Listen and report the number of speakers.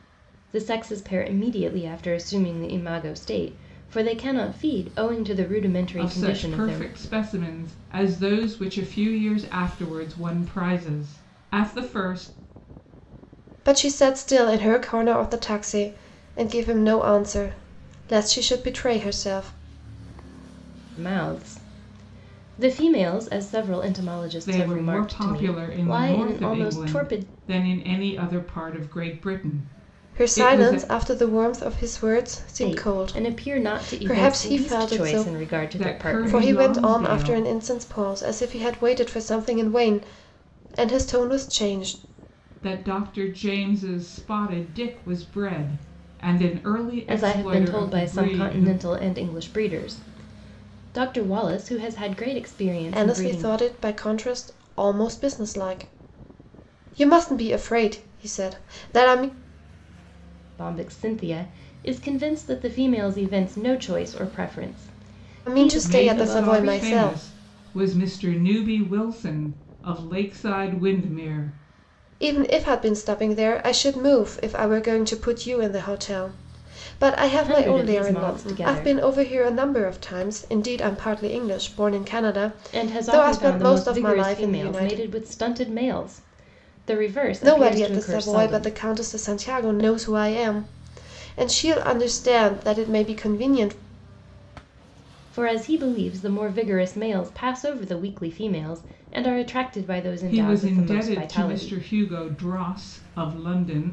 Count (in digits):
3